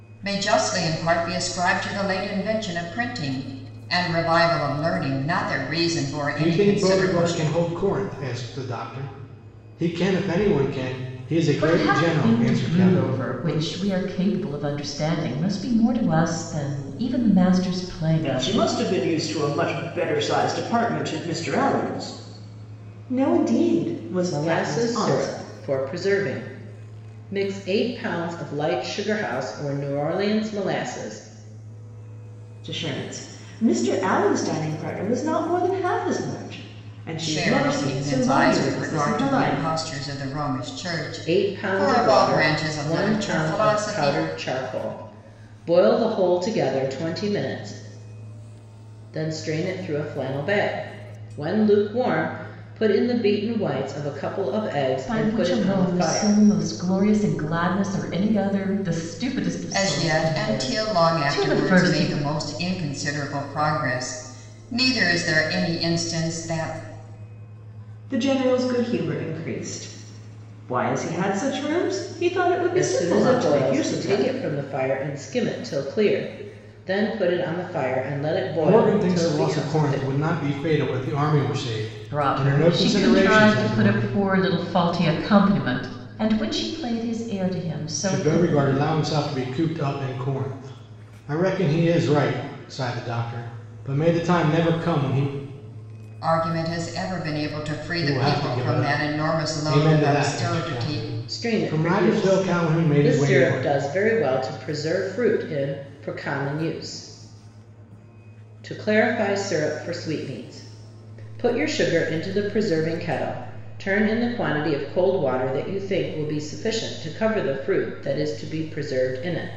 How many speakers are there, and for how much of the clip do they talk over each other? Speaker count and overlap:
5, about 22%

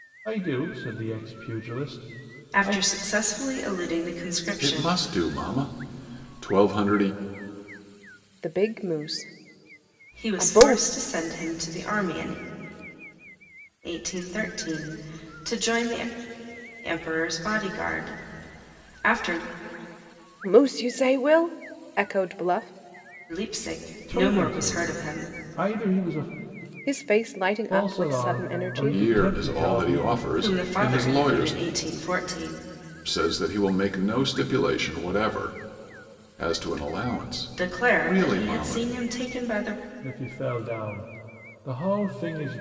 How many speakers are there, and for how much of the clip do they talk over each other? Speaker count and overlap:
4, about 19%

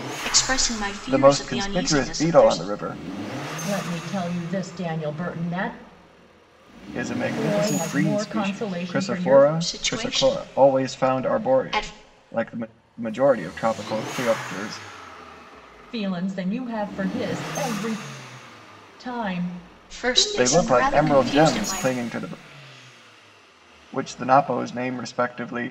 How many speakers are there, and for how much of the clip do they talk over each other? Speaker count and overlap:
3, about 31%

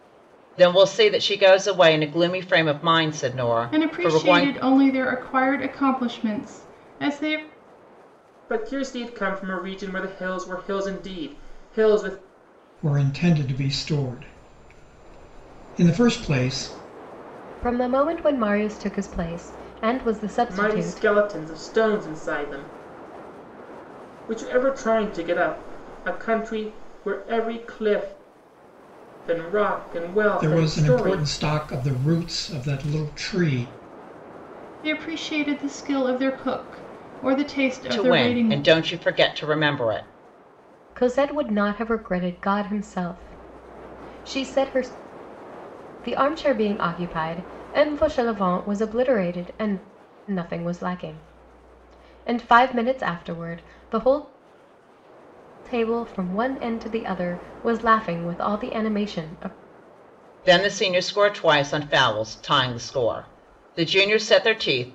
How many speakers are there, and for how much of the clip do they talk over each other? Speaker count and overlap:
5, about 5%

